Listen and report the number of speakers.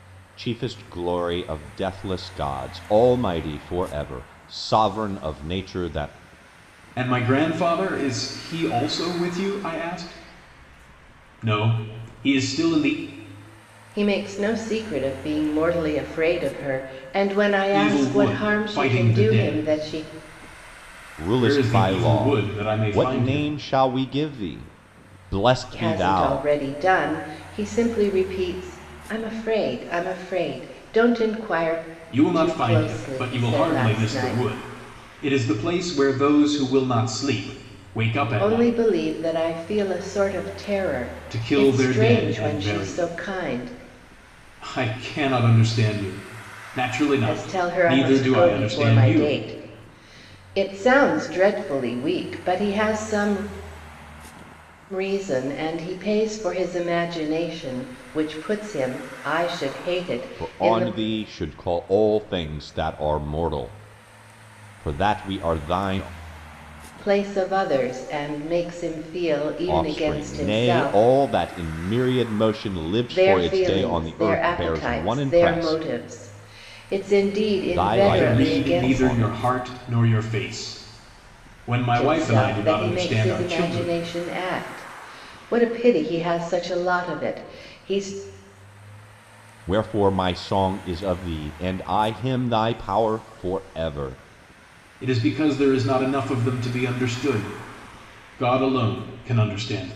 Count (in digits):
3